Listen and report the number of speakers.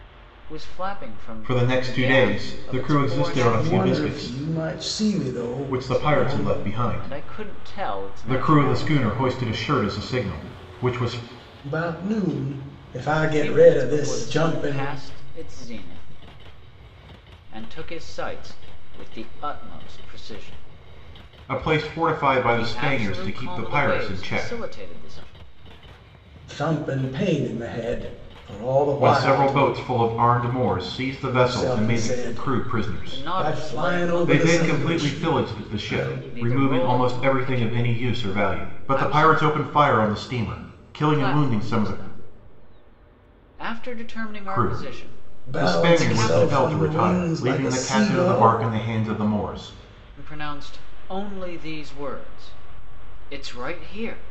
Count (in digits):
3